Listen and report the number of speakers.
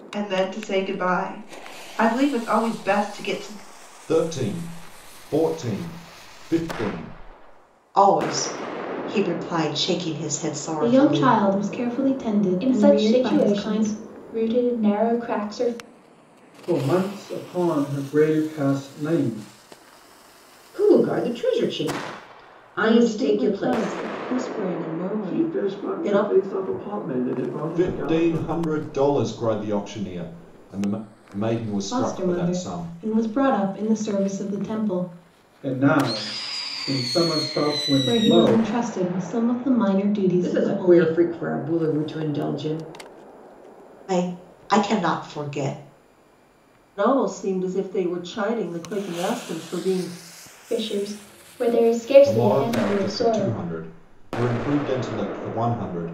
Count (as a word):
nine